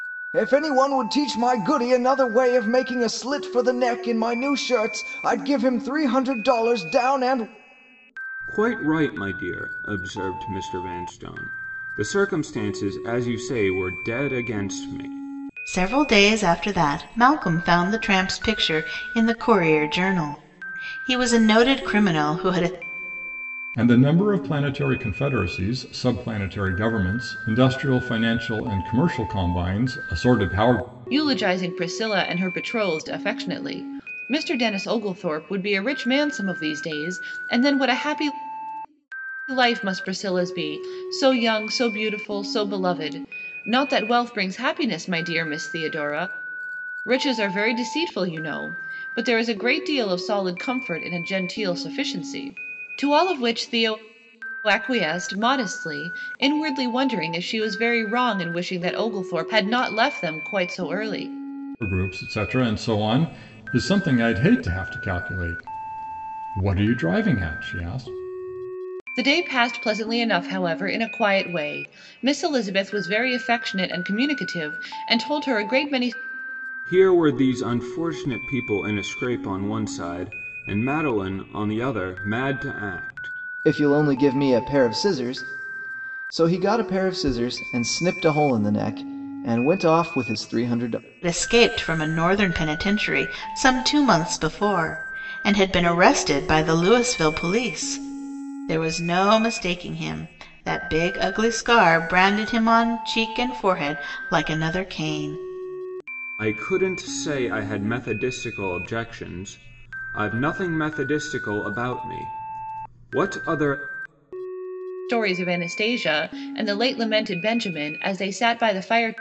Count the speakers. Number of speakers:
5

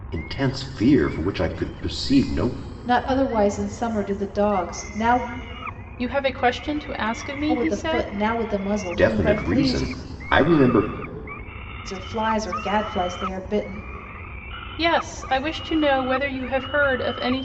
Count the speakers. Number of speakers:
3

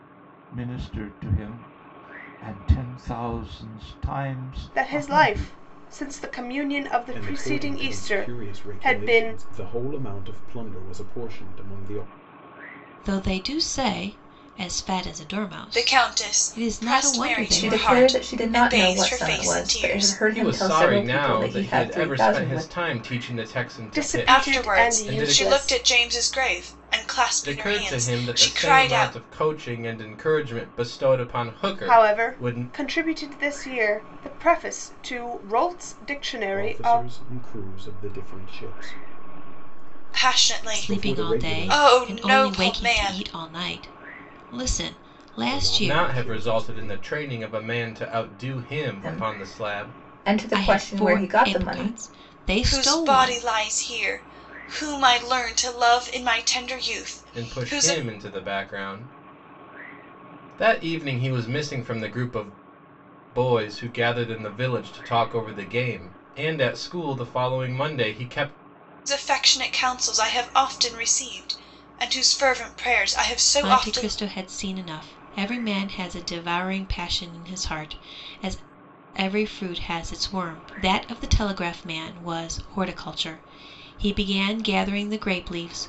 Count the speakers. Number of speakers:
7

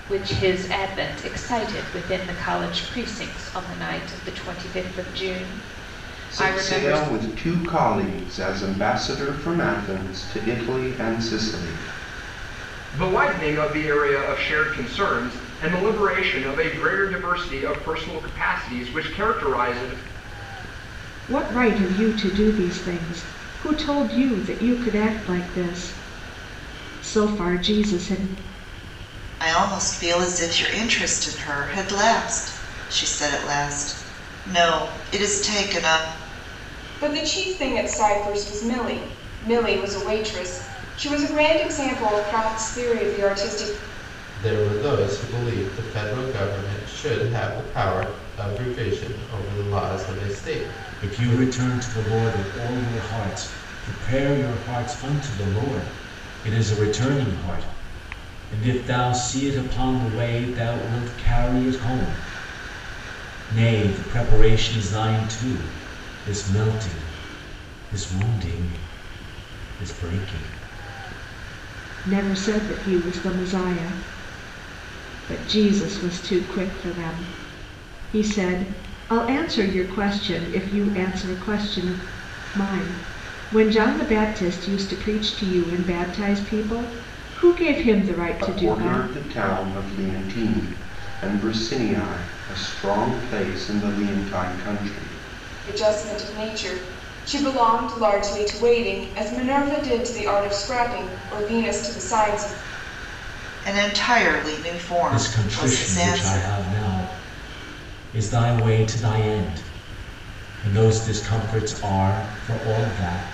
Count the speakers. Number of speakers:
8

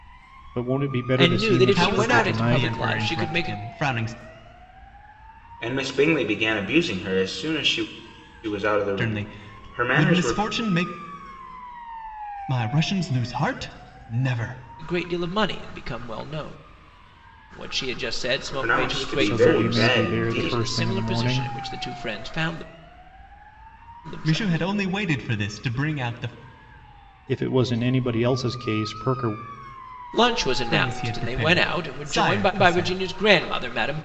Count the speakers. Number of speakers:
4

